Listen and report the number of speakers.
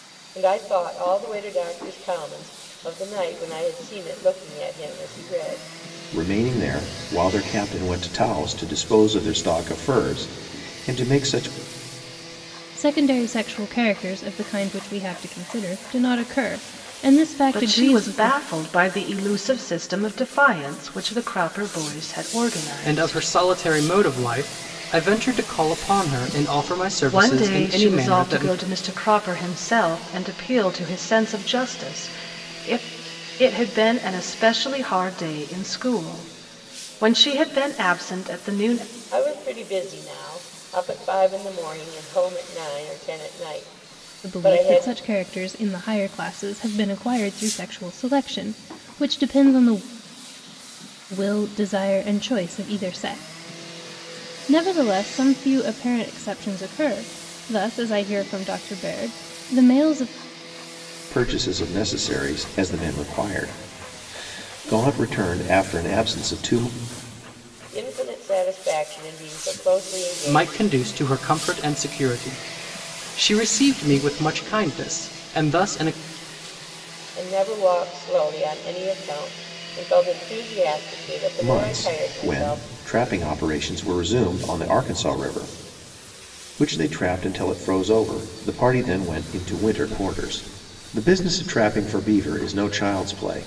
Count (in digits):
5